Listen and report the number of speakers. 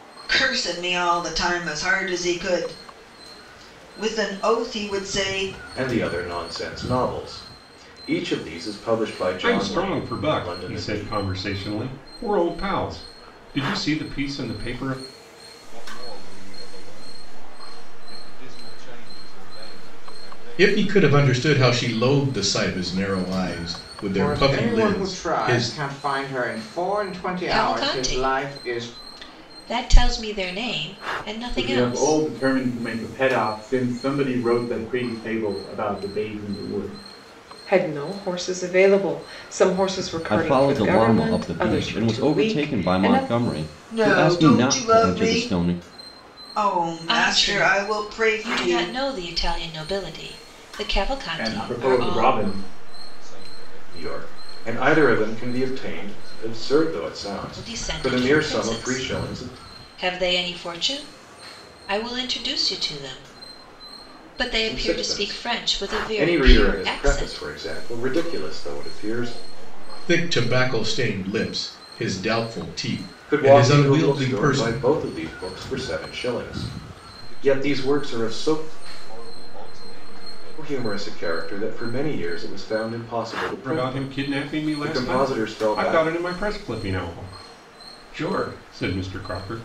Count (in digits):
10